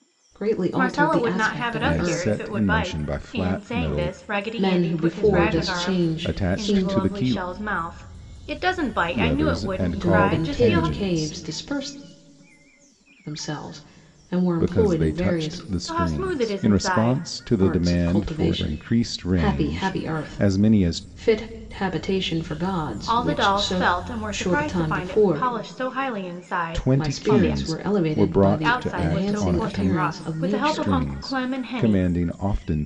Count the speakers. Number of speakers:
3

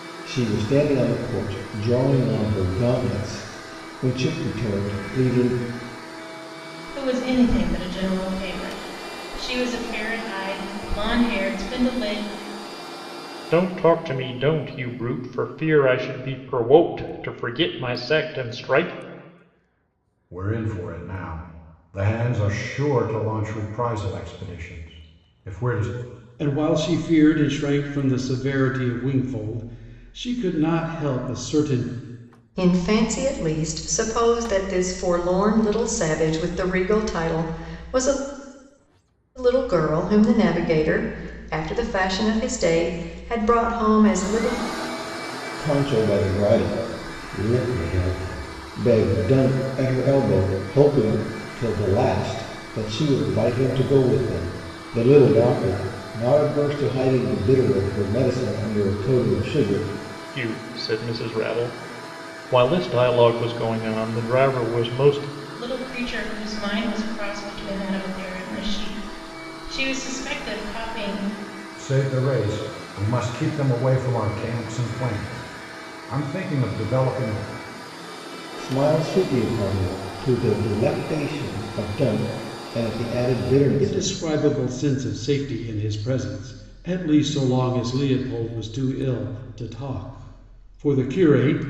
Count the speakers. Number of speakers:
6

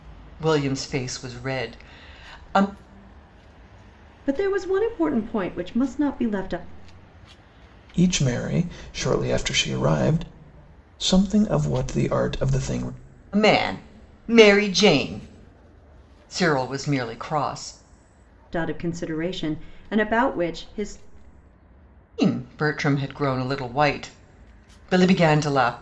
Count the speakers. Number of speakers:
3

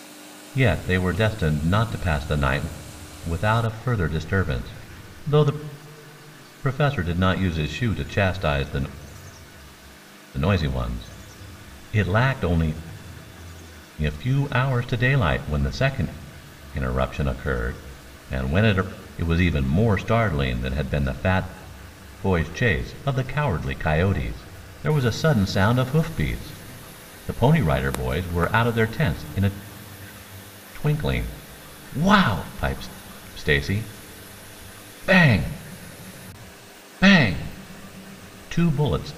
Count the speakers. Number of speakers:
1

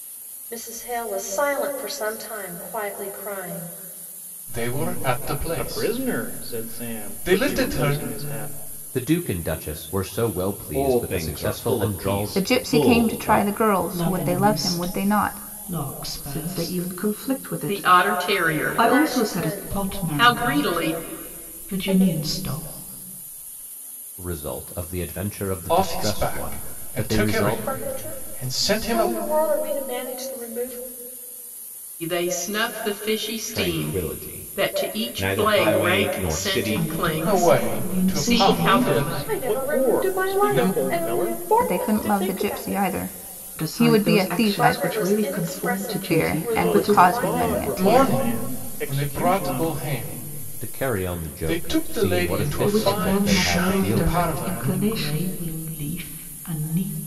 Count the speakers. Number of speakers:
9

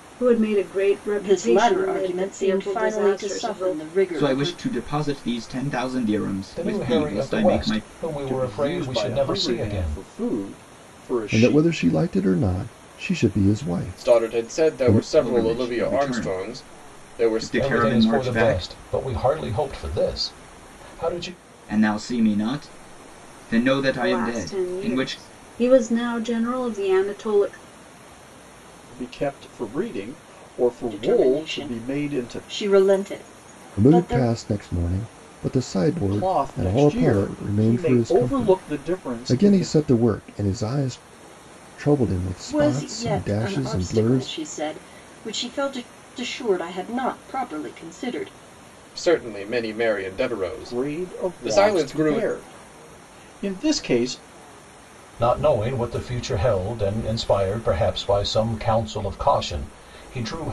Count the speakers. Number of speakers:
7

